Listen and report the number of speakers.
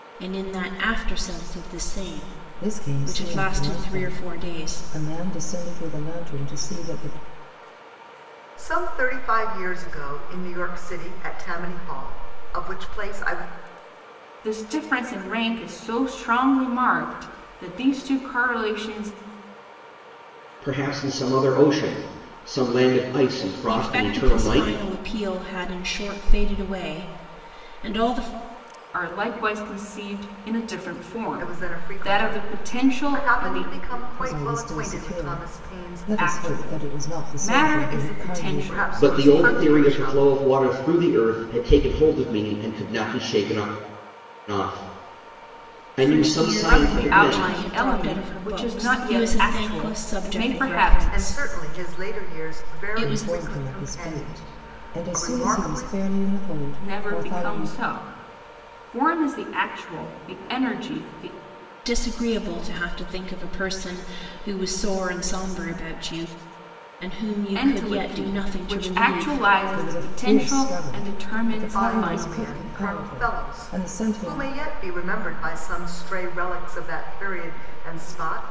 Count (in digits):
5